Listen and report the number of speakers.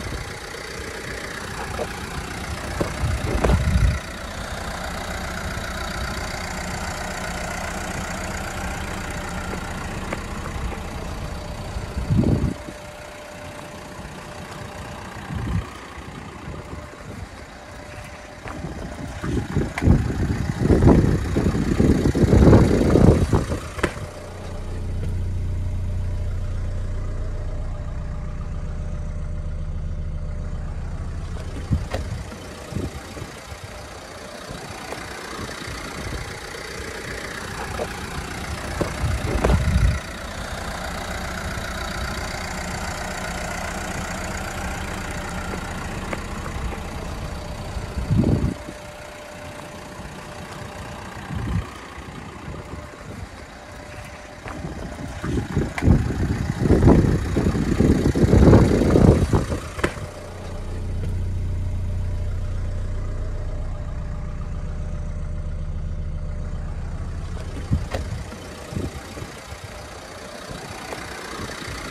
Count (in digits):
0